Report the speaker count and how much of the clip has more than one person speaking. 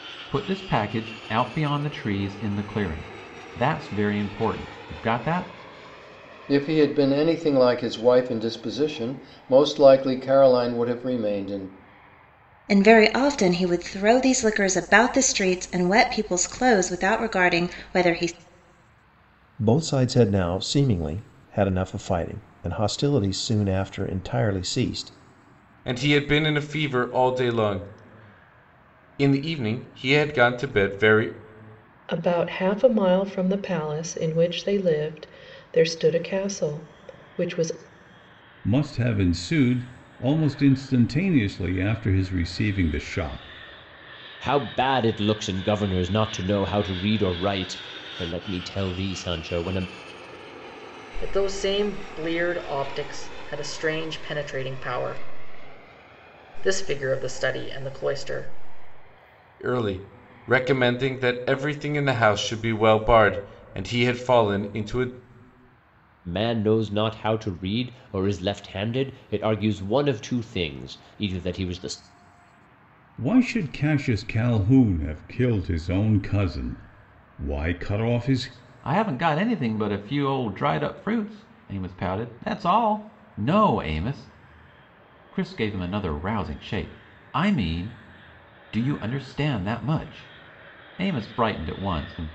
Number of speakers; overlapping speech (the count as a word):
nine, no overlap